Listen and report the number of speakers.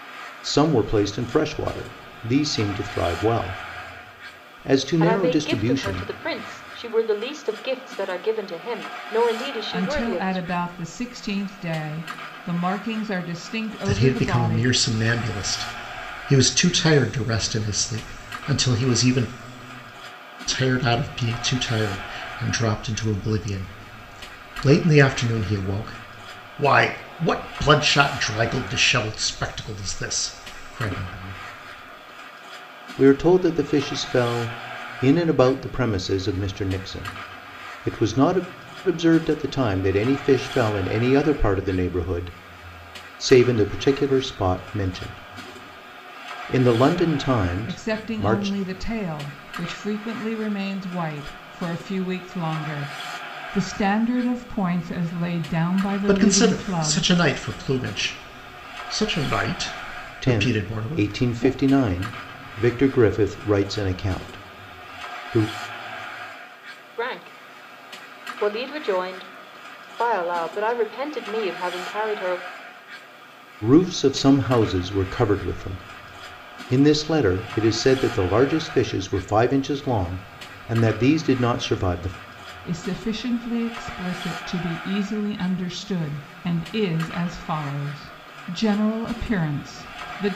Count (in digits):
4